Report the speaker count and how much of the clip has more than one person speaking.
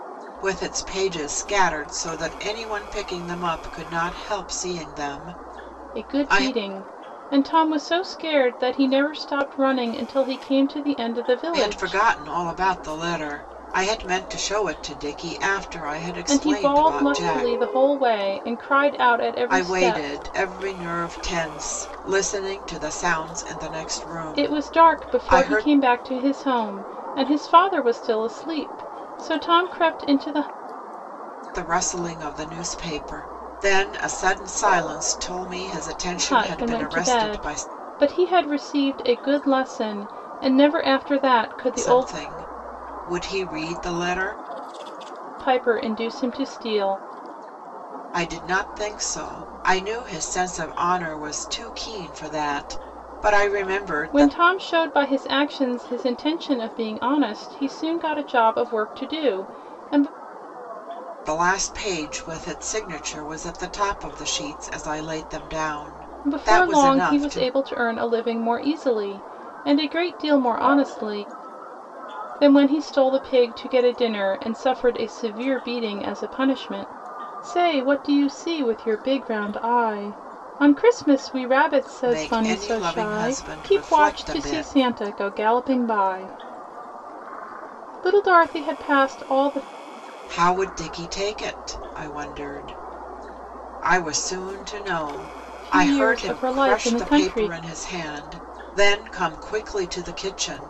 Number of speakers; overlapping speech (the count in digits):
2, about 12%